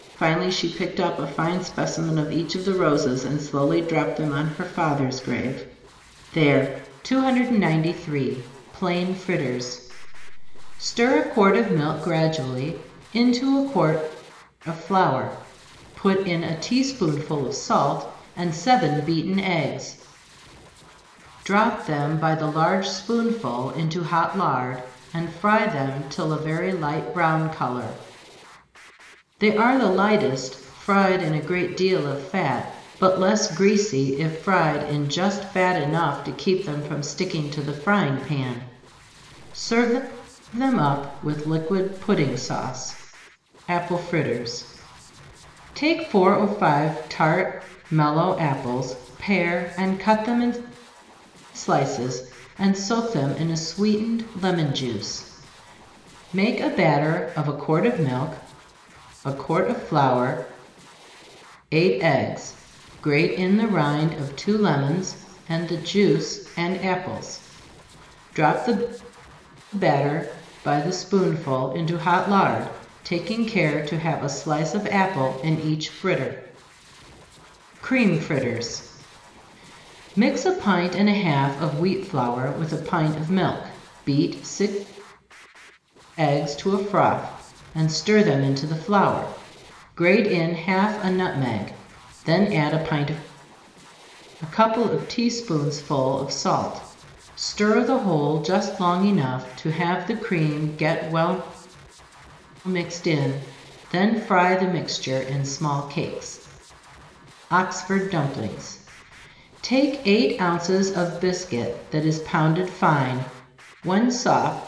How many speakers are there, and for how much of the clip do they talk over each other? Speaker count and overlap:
1, no overlap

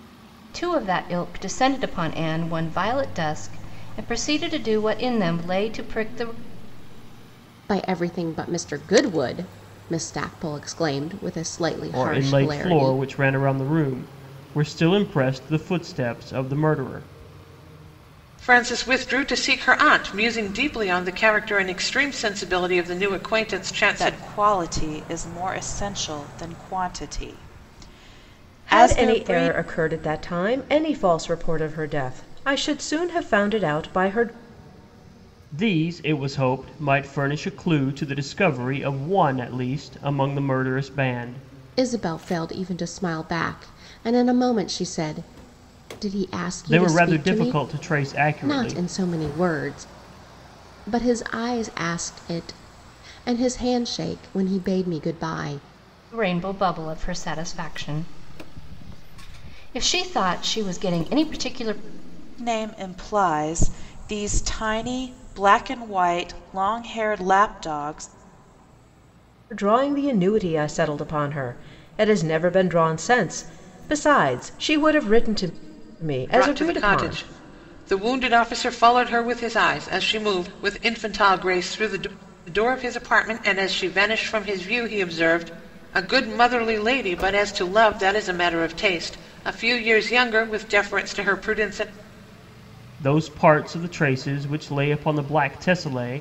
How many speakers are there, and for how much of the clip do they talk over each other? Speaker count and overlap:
6, about 5%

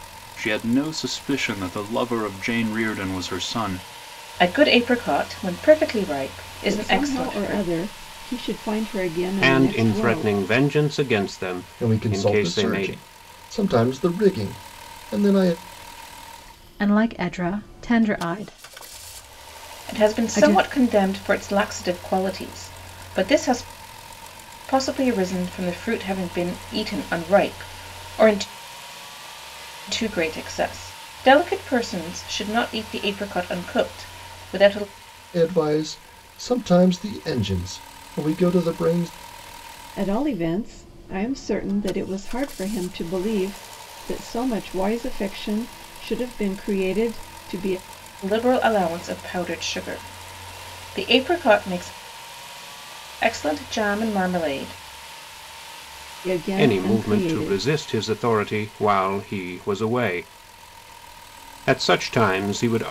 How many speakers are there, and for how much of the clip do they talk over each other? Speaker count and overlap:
6, about 8%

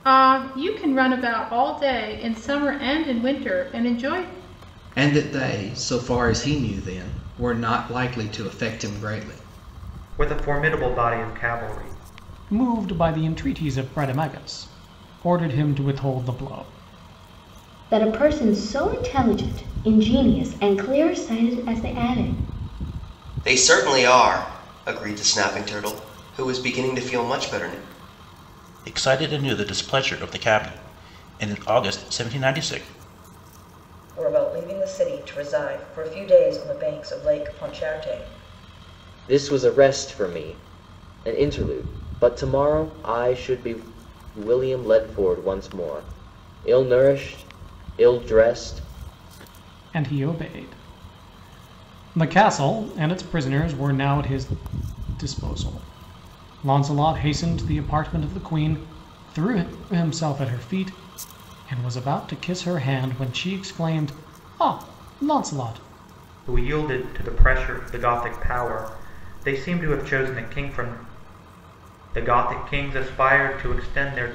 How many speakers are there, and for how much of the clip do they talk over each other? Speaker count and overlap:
9, no overlap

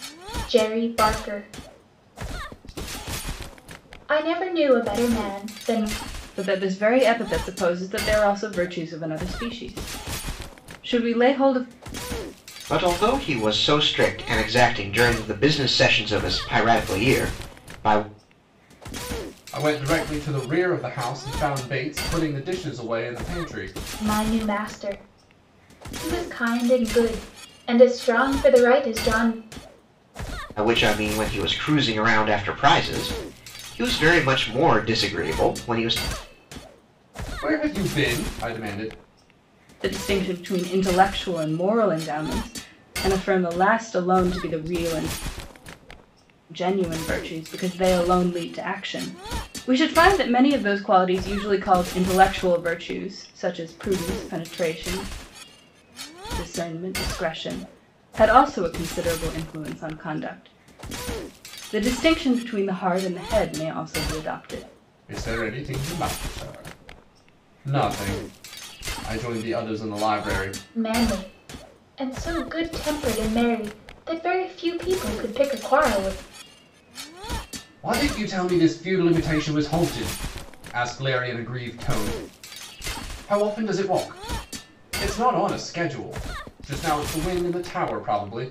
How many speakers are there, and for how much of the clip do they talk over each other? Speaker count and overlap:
4, no overlap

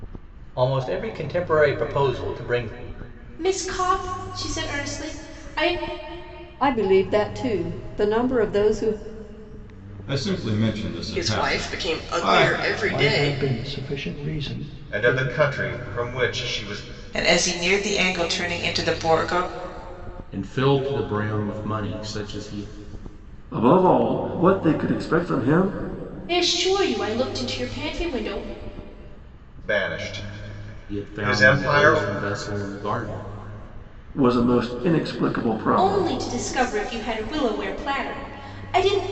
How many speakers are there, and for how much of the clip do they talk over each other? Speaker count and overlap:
10, about 10%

